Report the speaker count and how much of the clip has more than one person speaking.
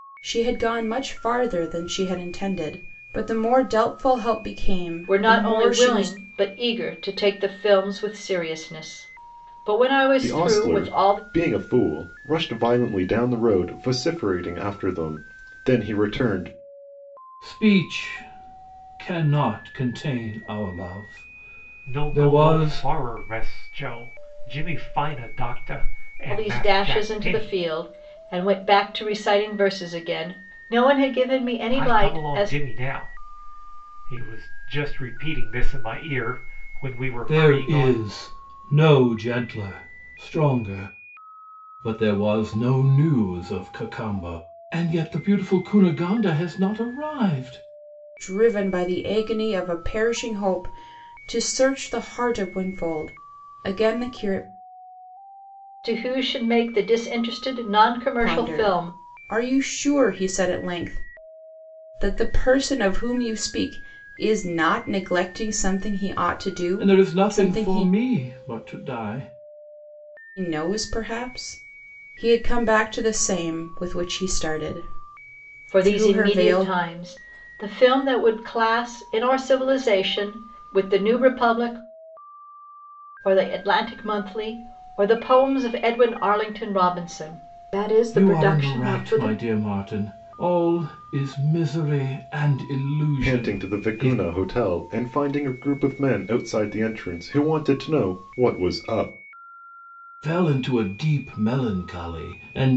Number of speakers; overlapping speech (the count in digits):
5, about 11%